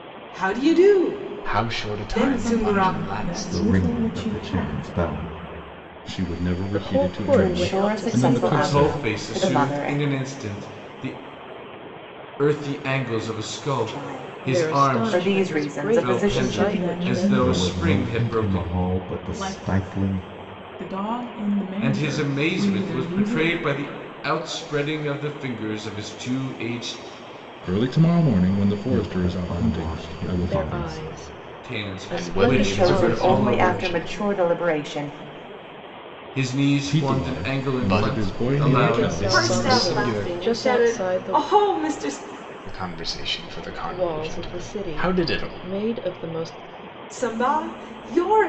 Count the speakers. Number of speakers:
8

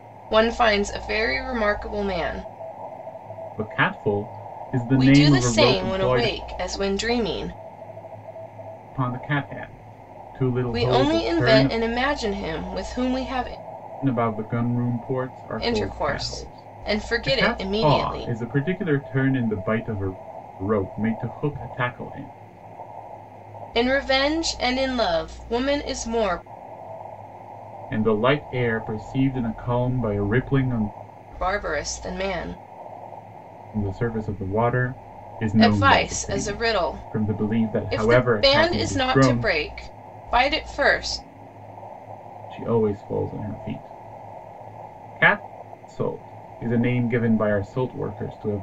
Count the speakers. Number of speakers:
2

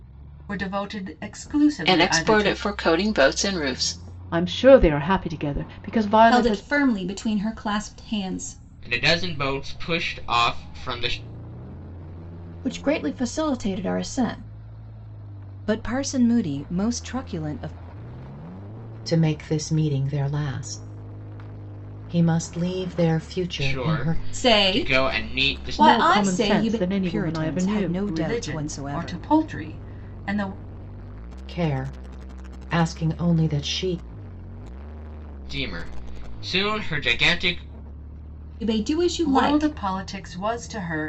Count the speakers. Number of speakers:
8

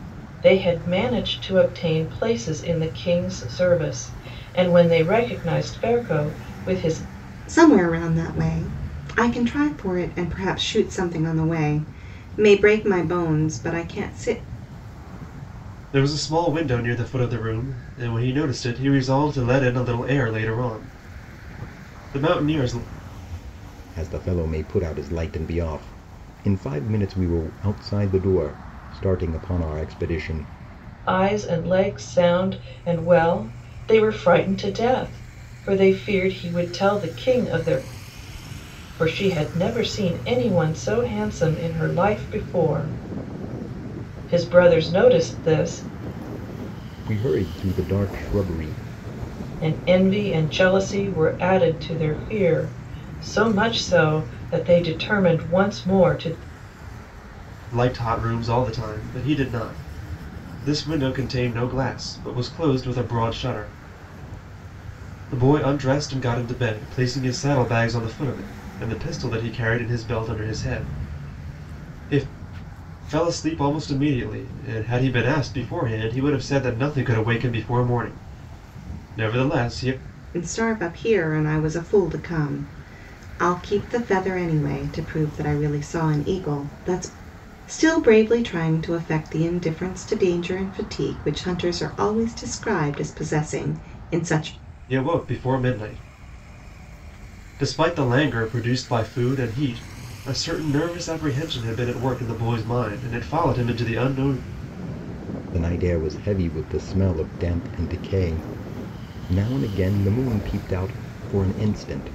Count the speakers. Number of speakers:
4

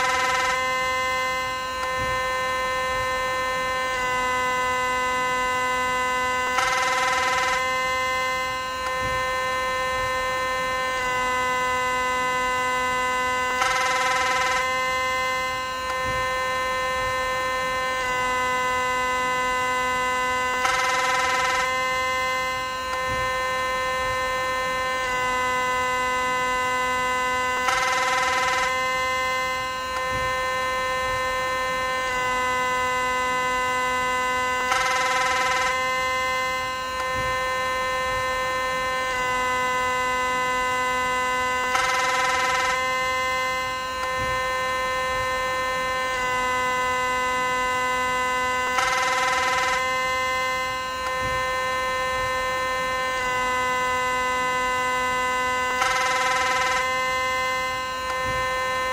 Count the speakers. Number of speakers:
0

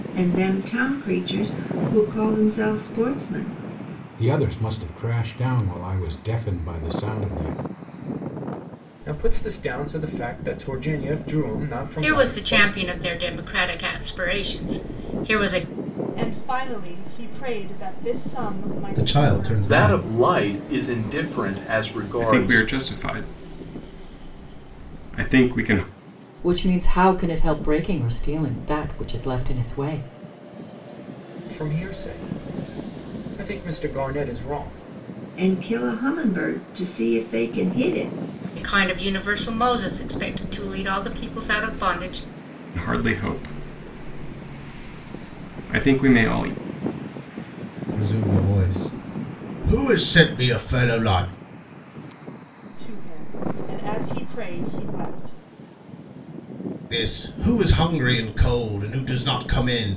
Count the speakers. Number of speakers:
9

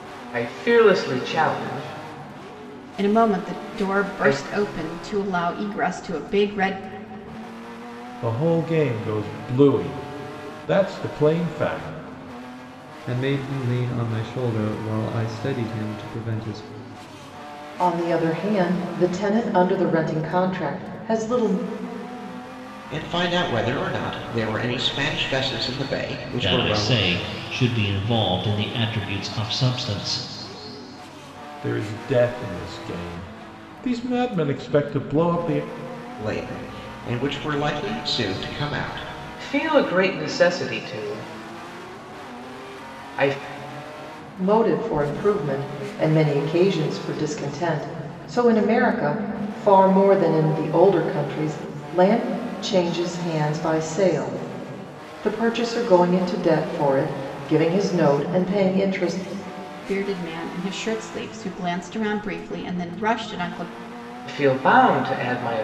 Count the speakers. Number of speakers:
7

